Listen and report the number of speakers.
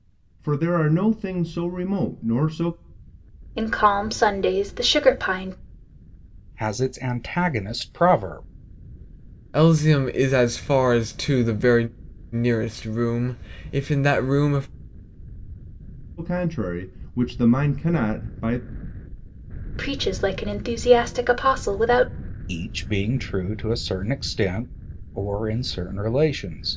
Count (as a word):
four